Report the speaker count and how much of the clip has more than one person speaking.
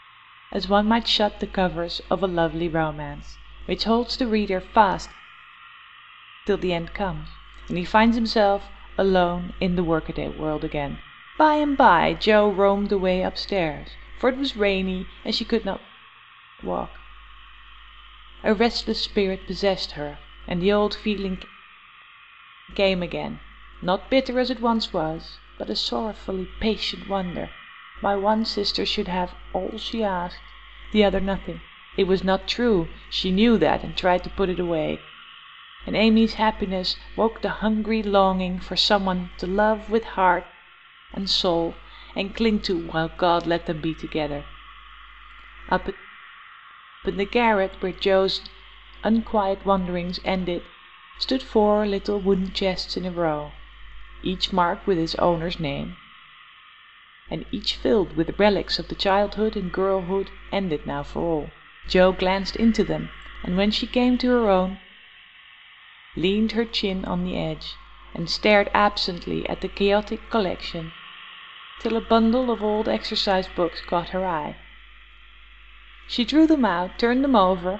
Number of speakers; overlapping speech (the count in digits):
1, no overlap